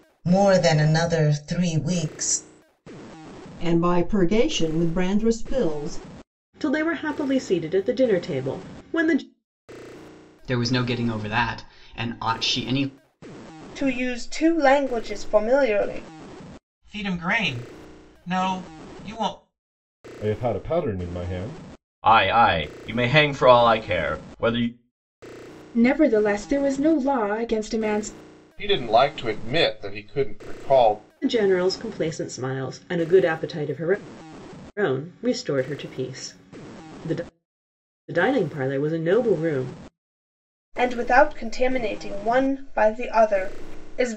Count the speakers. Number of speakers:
ten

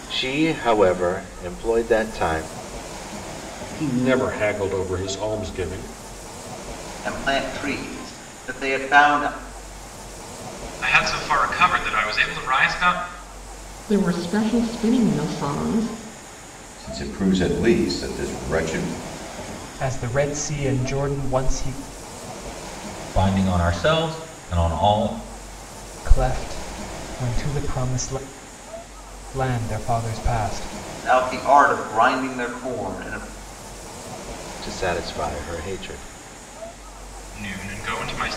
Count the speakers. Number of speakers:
eight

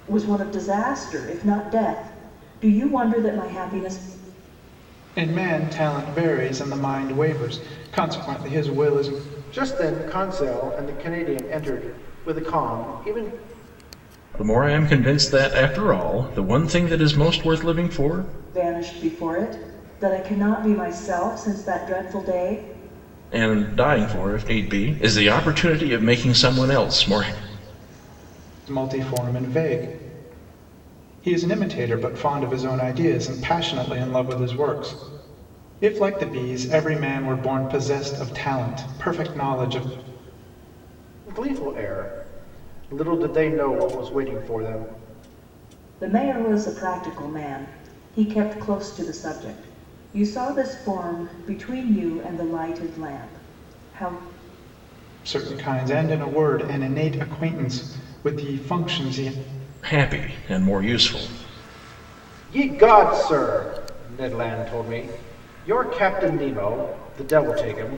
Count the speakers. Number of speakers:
four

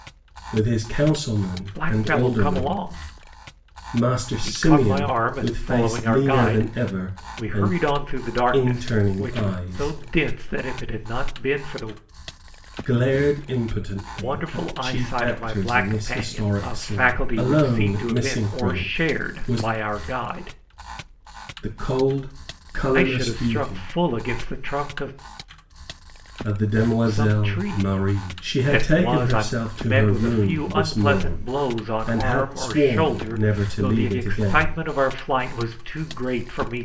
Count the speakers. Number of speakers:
two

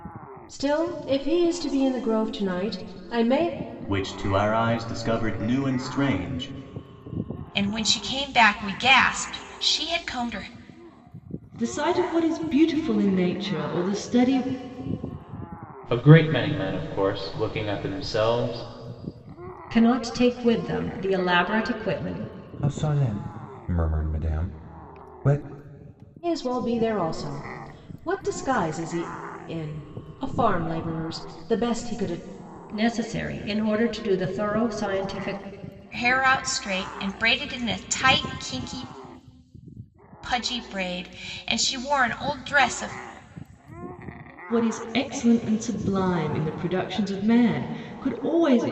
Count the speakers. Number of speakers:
seven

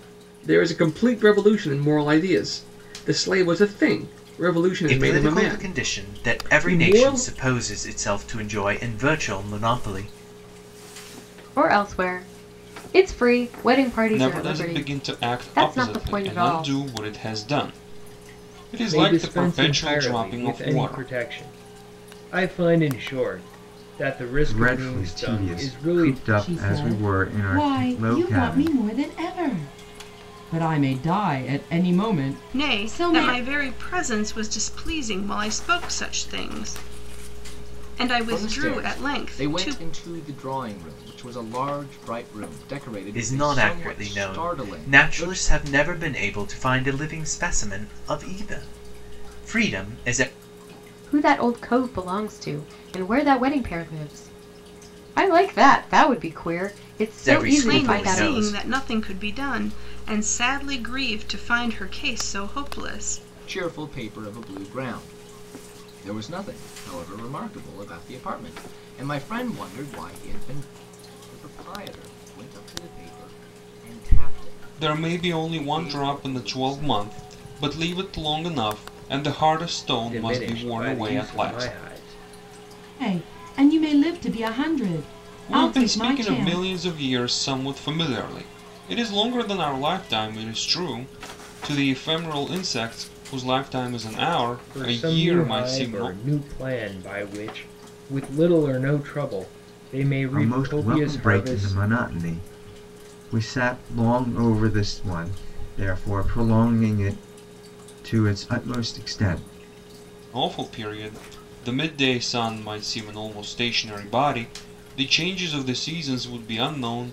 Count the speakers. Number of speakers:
nine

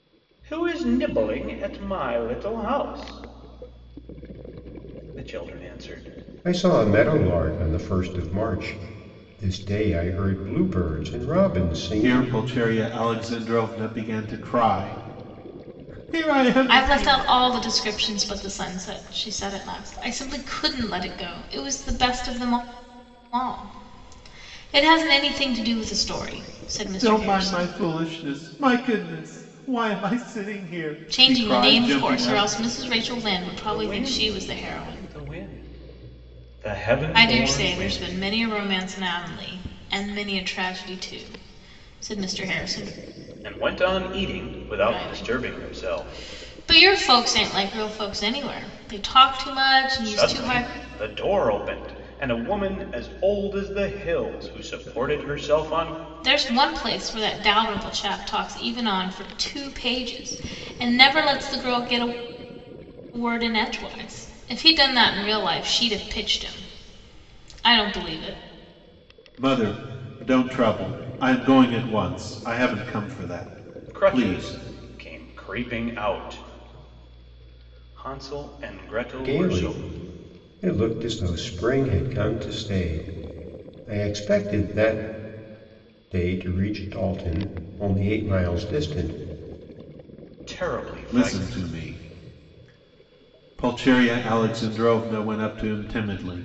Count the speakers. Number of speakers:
four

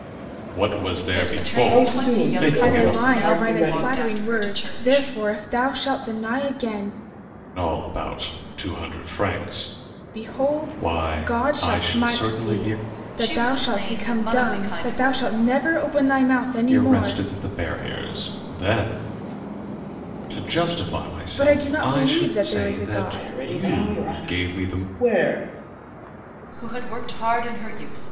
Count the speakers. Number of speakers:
four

